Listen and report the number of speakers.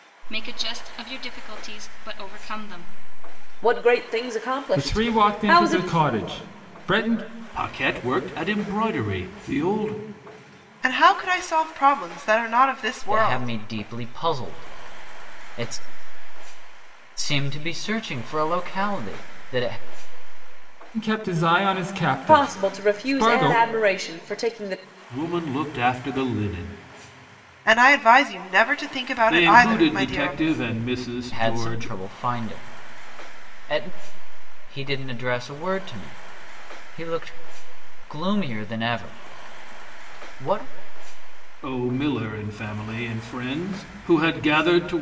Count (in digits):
6